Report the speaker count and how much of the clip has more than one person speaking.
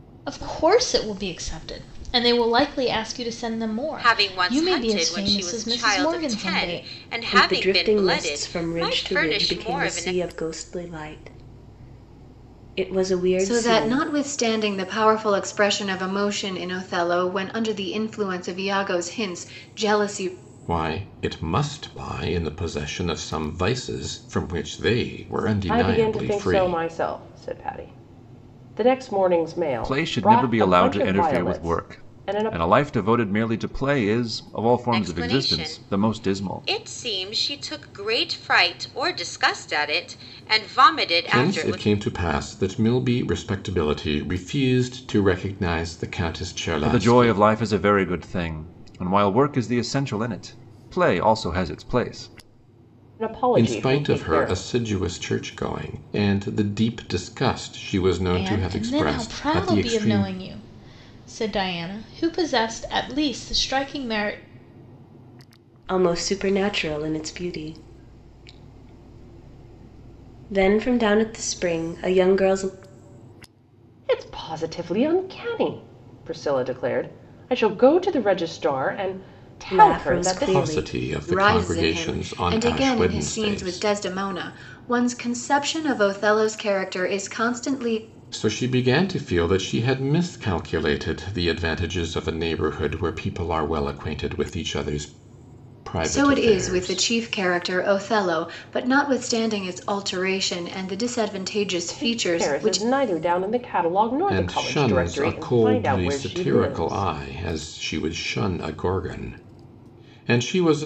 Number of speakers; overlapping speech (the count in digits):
7, about 23%